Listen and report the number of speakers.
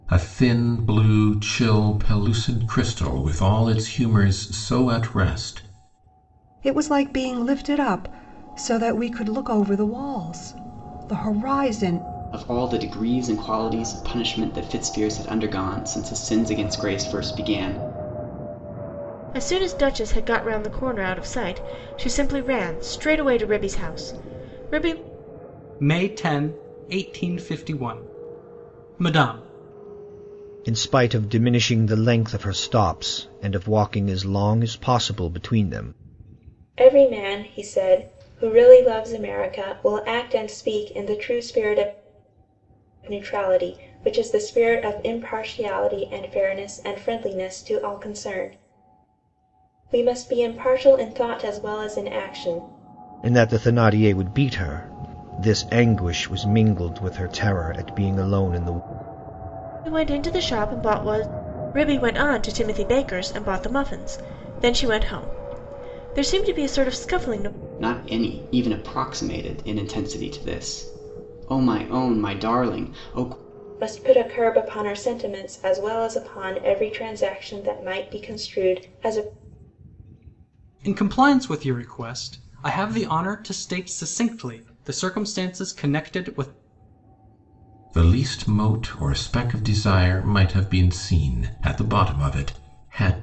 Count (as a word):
seven